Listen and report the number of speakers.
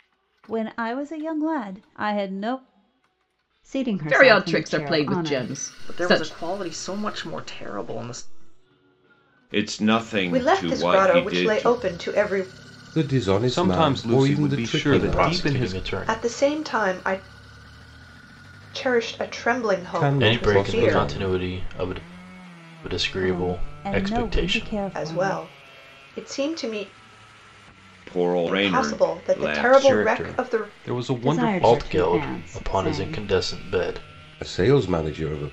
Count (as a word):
nine